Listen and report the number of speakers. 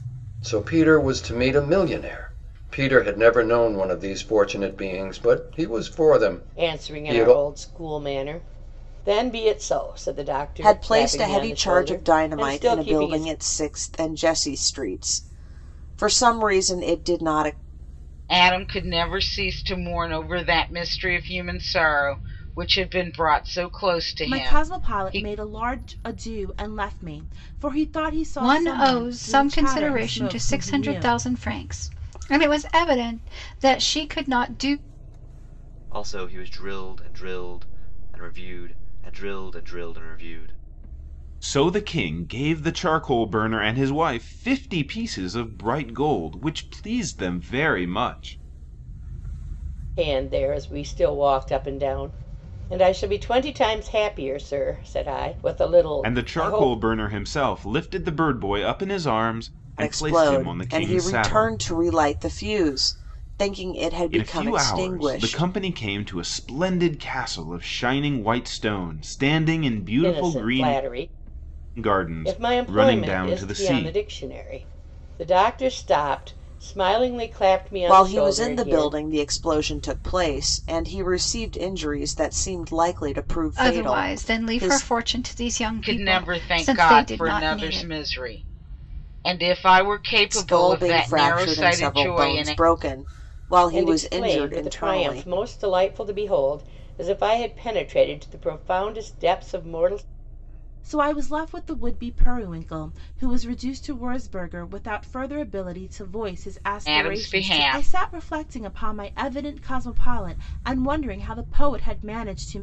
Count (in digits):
8